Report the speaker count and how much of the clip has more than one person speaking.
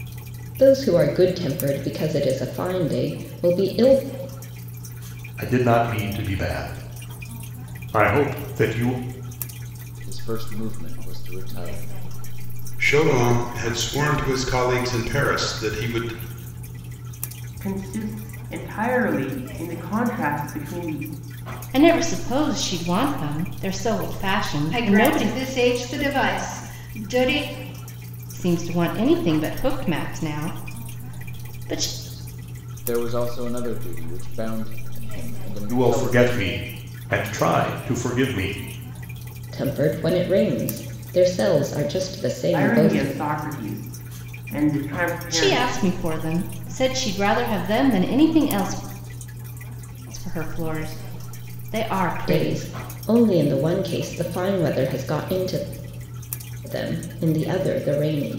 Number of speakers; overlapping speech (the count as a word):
seven, about 6%